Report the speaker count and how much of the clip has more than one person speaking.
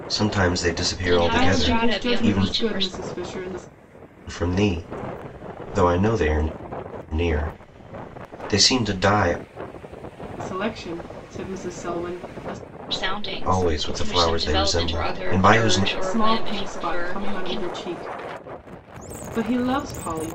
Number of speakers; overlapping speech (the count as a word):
three, about 30%